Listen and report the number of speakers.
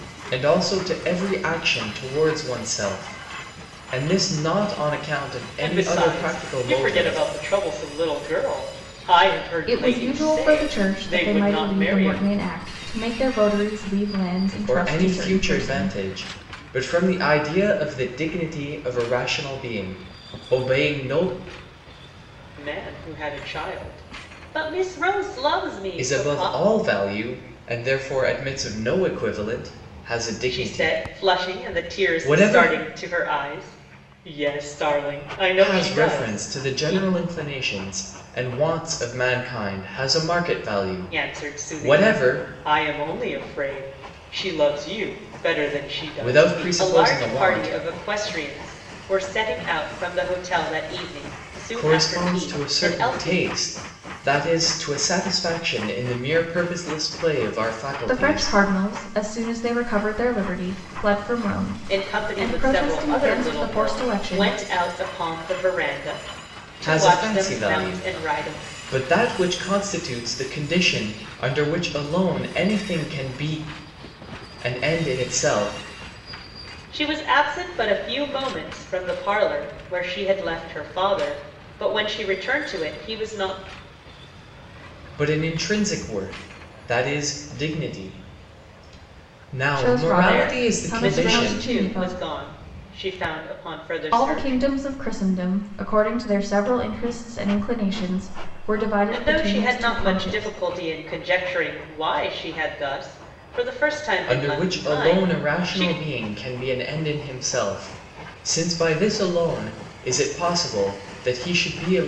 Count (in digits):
3